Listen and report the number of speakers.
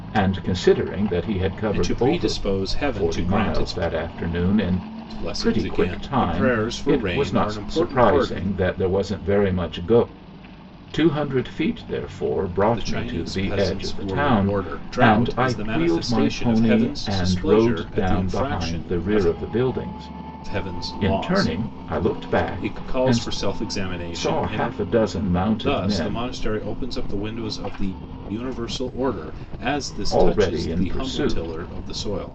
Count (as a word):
two